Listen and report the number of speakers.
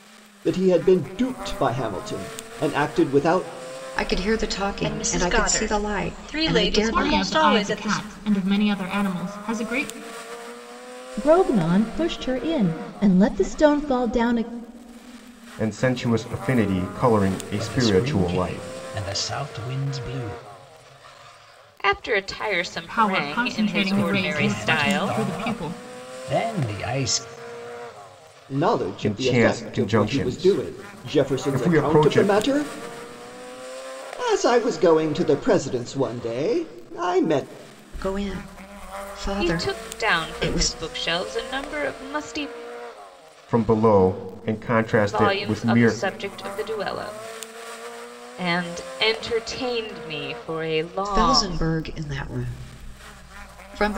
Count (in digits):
8